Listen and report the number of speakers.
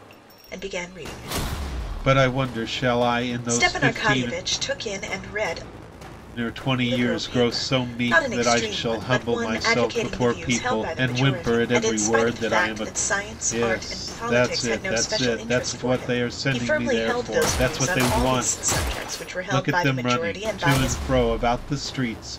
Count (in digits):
2